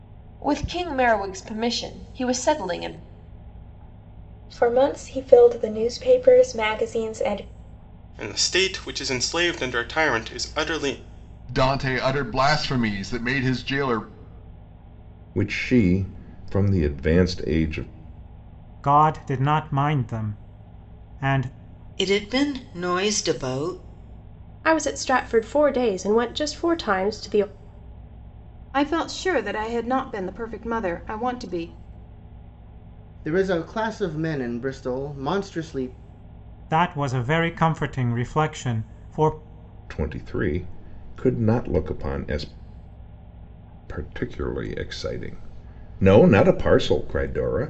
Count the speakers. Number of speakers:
10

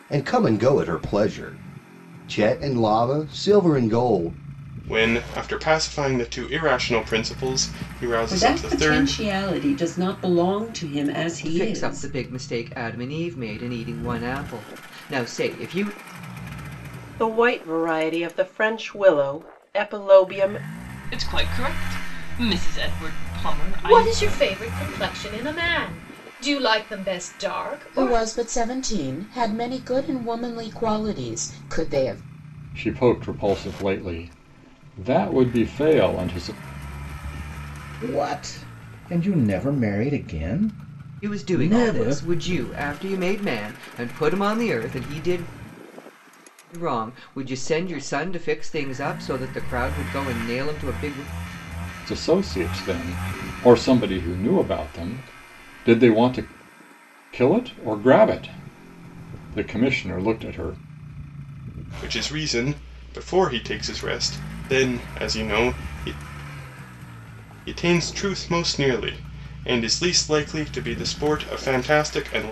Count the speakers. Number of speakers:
10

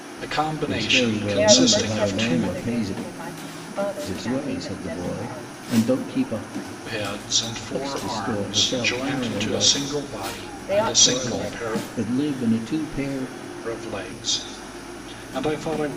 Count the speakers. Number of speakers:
3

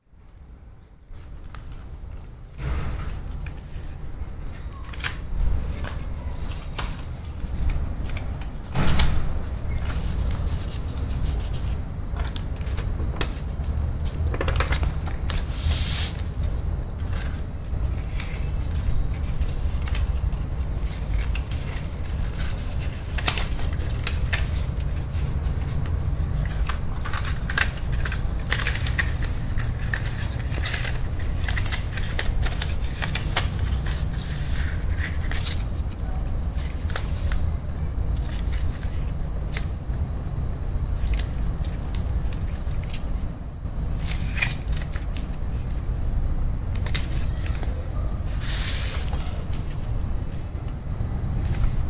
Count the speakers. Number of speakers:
0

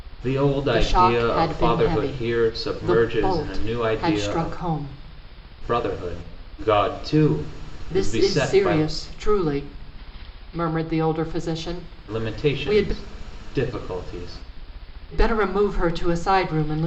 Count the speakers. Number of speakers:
2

